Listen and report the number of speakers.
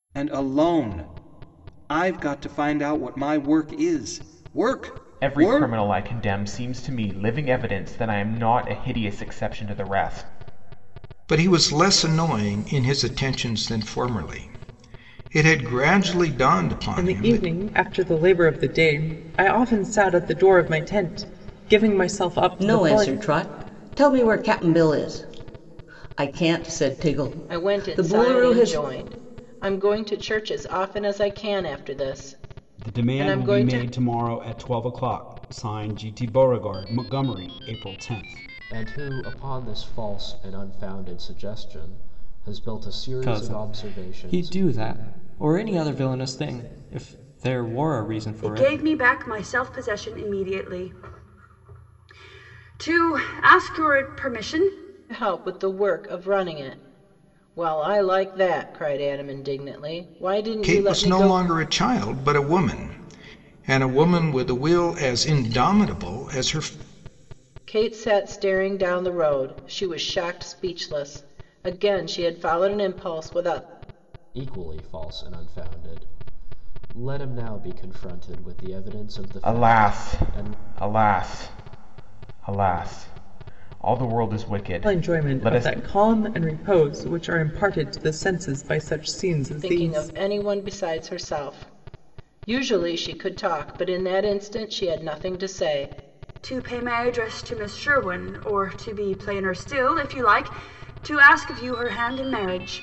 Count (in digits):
10